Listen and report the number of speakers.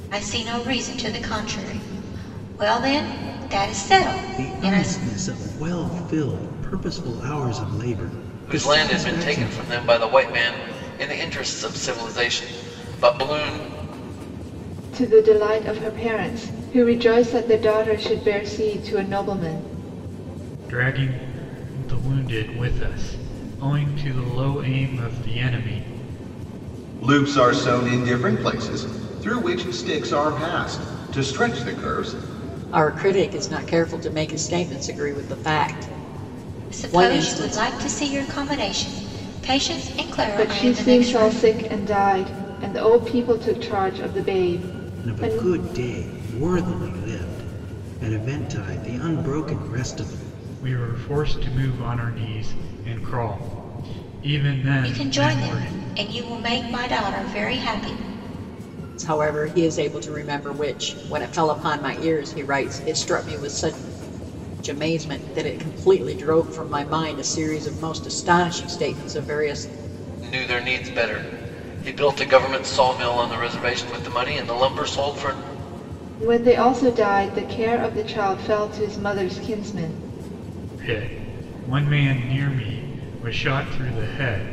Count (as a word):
seven